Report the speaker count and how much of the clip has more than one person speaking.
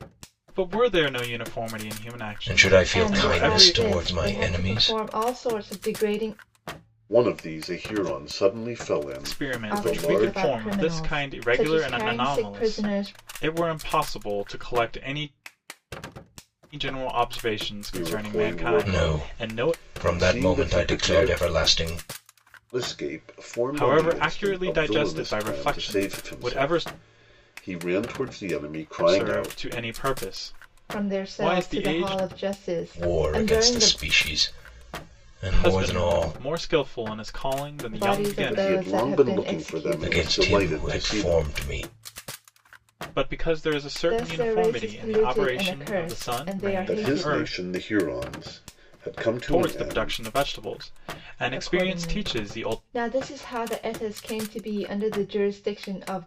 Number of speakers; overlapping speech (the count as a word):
four, about 47%